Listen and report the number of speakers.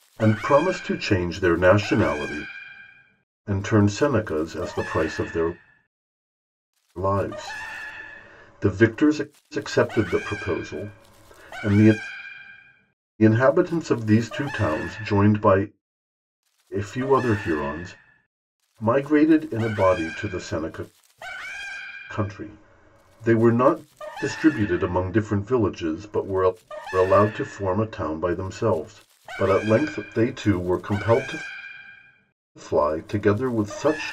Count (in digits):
1